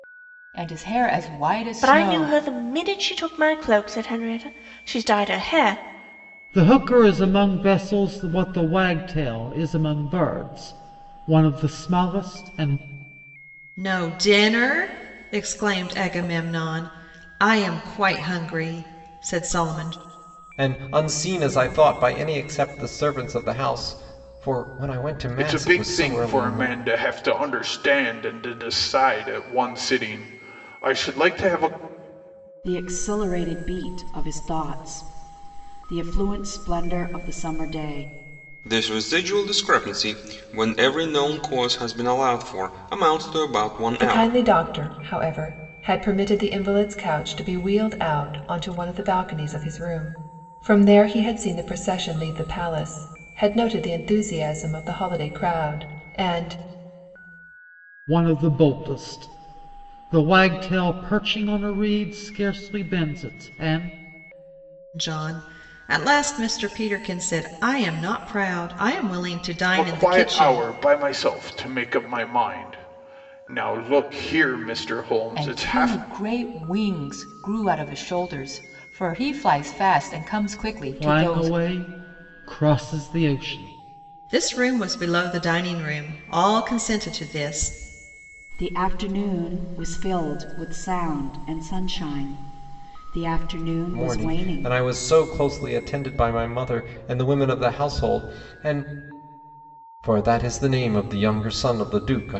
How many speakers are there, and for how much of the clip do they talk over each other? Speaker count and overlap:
9, about 5%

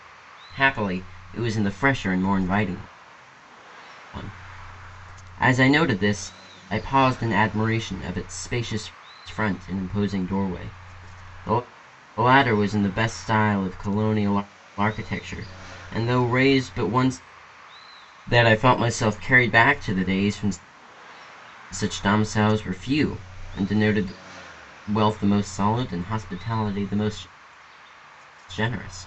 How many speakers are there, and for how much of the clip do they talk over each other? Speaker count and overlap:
1, no overlap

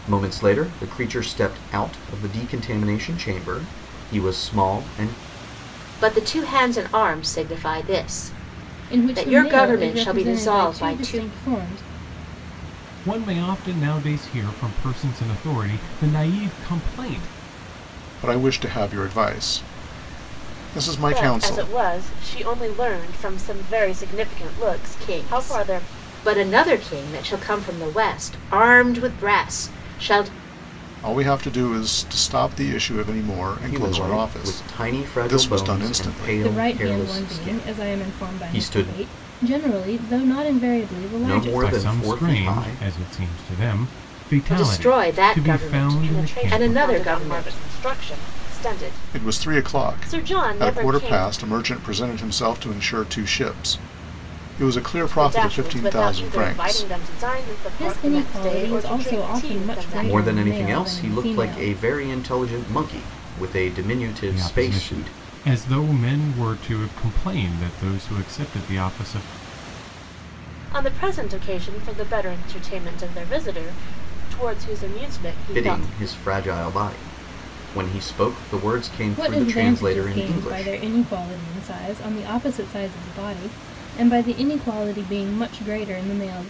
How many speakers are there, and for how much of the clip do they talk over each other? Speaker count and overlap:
6, about 29%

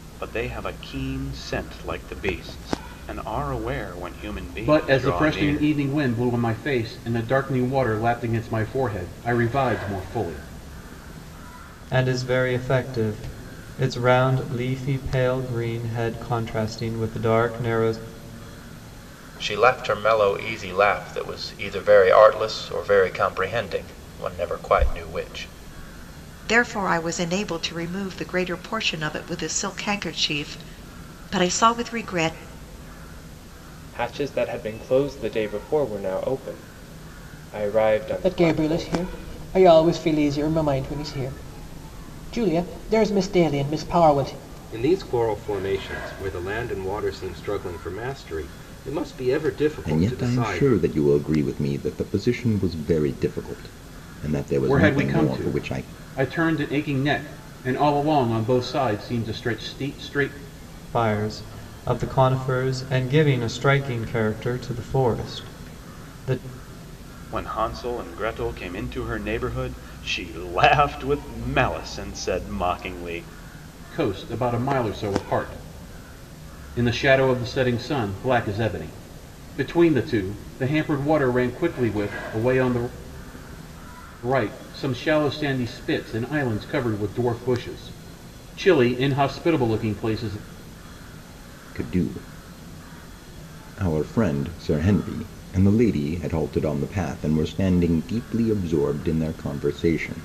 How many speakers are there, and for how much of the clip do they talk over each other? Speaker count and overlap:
9, about 4%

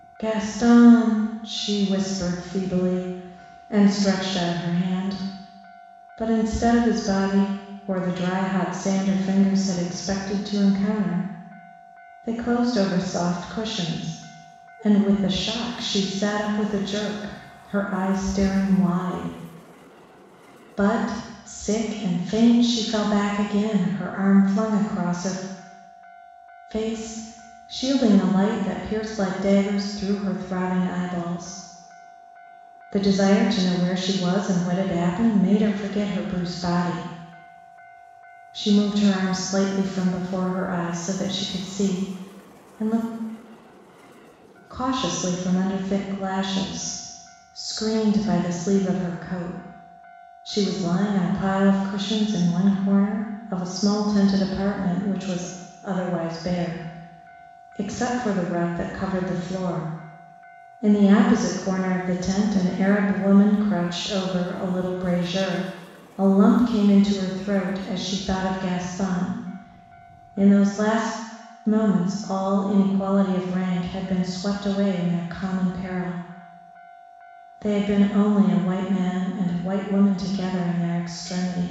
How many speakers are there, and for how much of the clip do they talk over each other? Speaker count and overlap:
1, no overlap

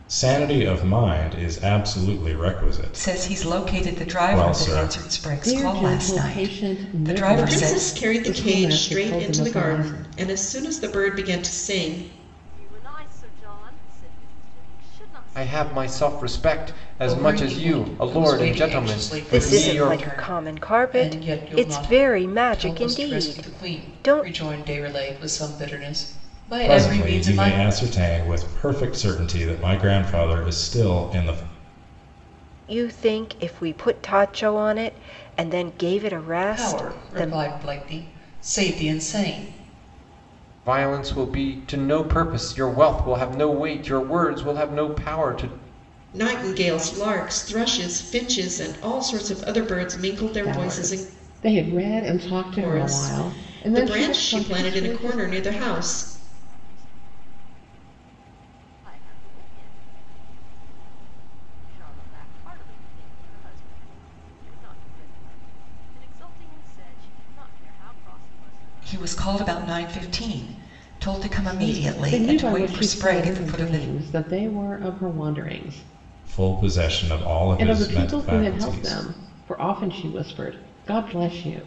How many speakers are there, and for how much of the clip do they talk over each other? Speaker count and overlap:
8, about 32%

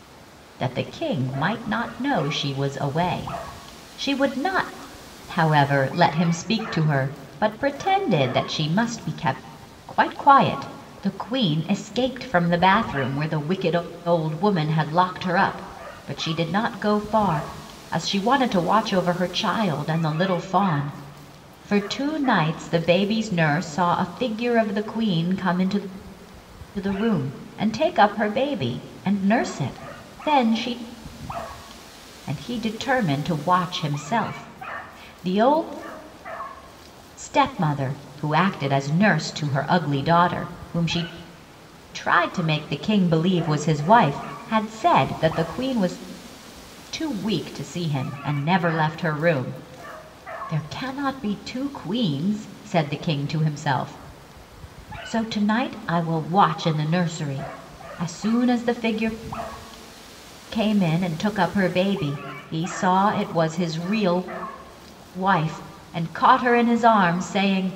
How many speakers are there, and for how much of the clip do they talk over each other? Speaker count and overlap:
1, no overlap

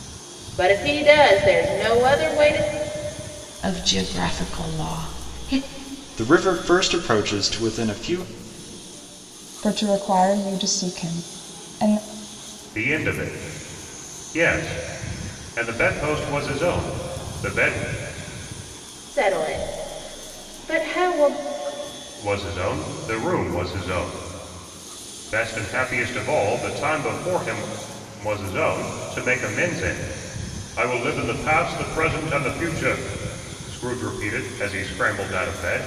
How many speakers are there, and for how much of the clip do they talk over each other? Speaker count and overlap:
5, no overlap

